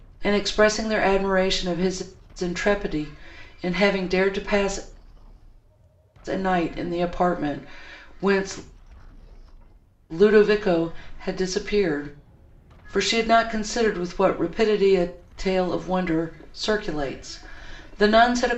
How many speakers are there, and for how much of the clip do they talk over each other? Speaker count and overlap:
1, no overlap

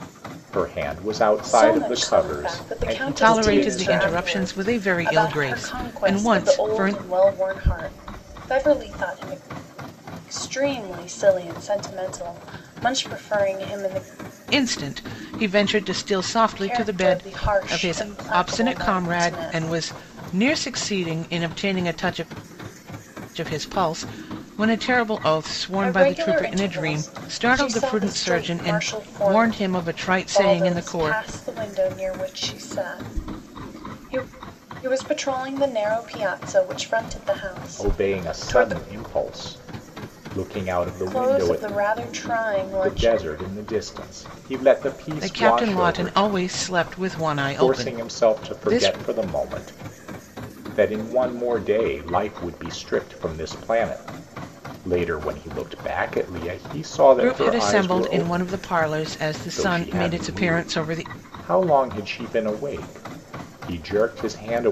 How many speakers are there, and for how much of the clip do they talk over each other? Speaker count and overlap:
3, about 33%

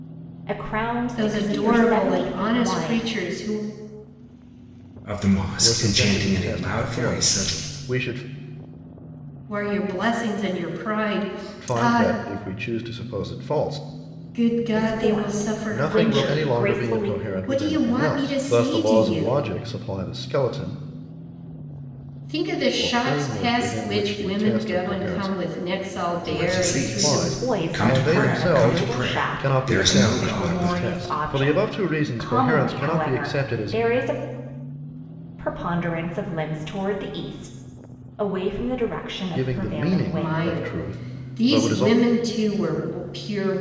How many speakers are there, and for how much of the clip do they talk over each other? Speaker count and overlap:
4, about 49%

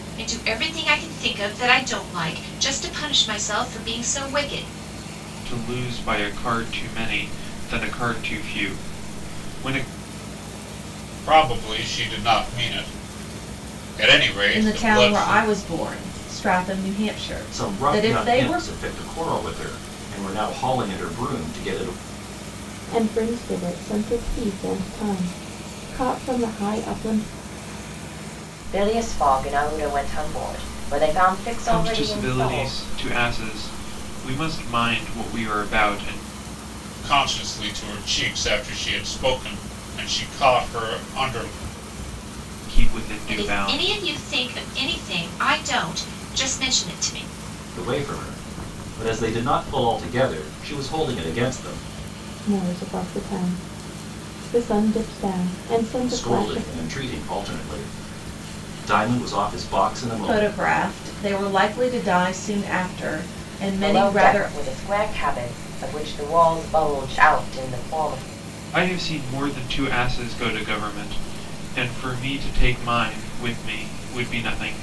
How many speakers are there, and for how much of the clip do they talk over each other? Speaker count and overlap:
7, about 8%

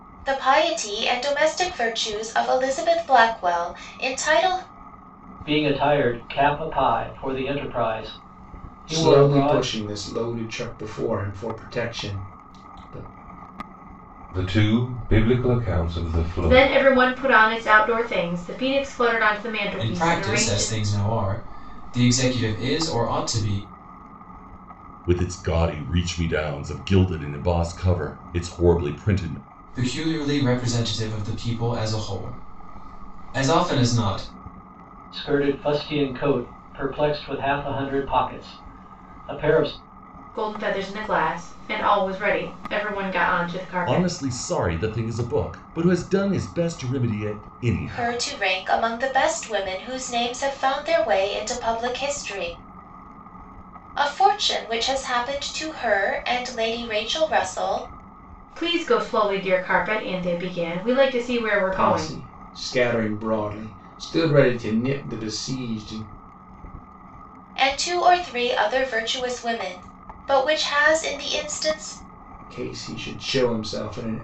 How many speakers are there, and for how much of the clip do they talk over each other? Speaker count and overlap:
7, about 5%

